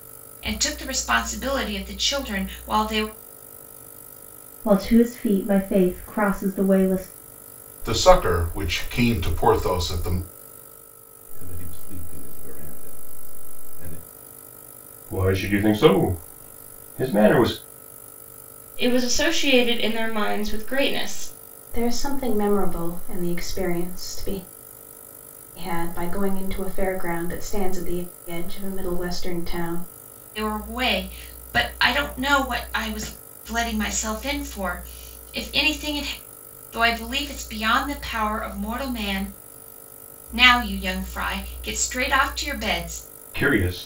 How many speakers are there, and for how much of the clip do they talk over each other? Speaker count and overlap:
7, no overlap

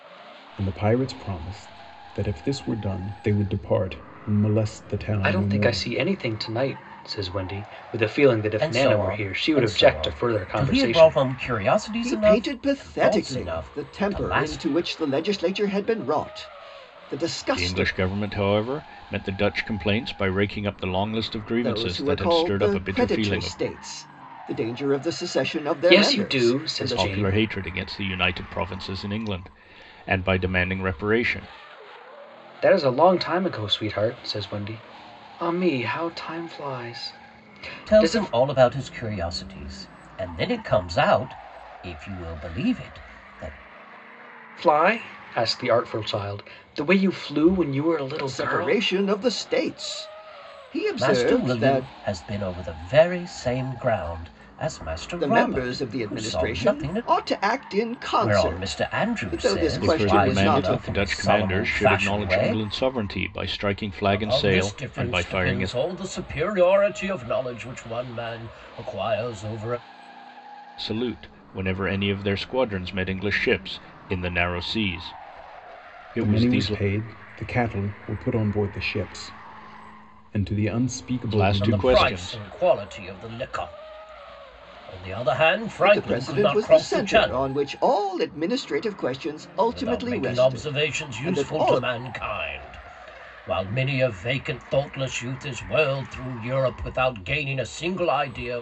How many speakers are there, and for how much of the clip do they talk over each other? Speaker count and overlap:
5, about 27%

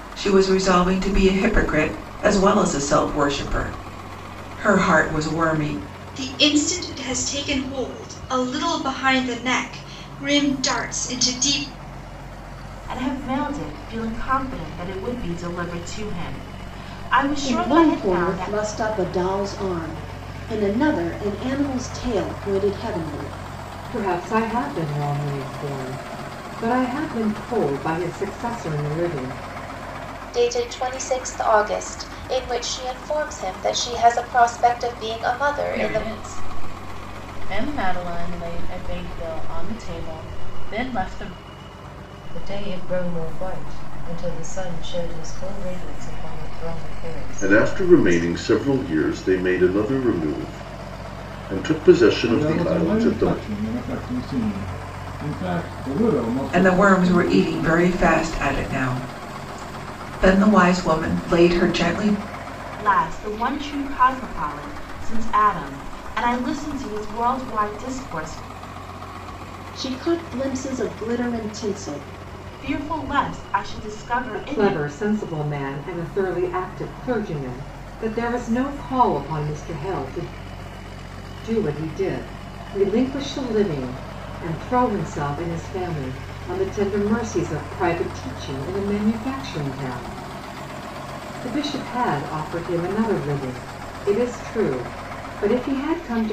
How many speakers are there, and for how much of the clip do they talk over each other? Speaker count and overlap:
10, about 6%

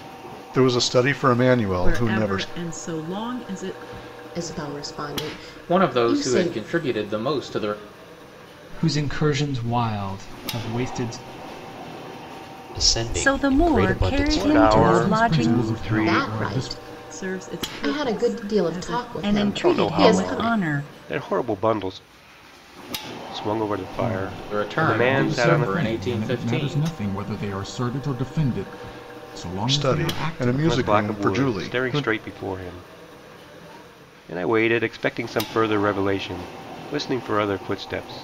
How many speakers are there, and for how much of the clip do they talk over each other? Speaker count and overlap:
9, about 37%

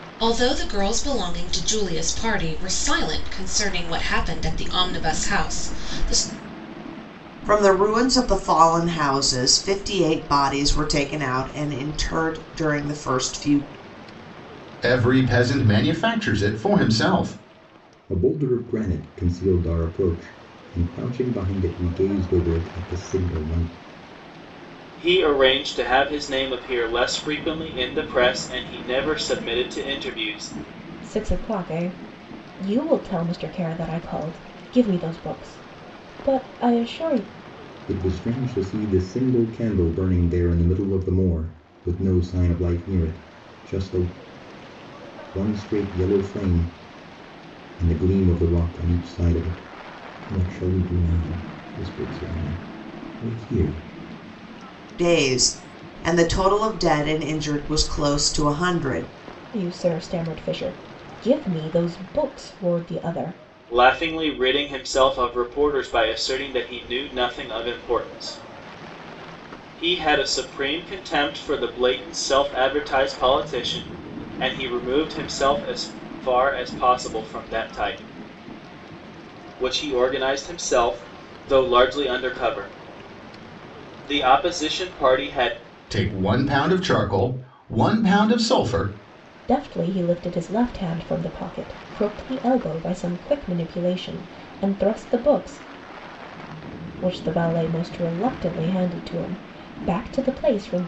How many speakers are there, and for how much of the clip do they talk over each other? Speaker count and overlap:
6, no overlap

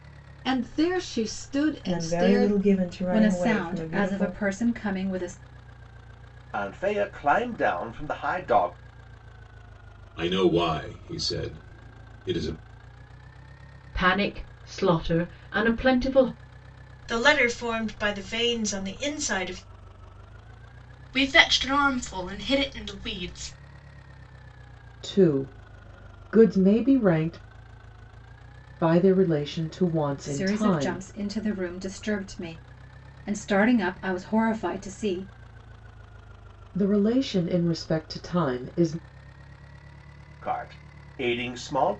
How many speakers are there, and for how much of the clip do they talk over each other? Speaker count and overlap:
9, about 7%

